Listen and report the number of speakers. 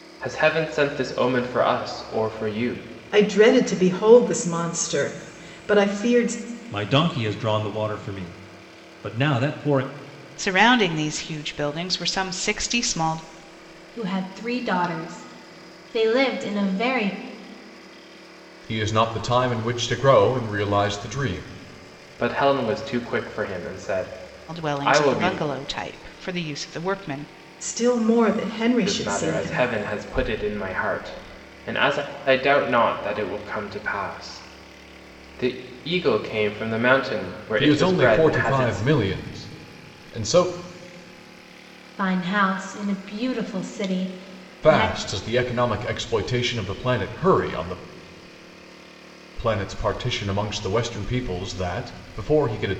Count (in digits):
6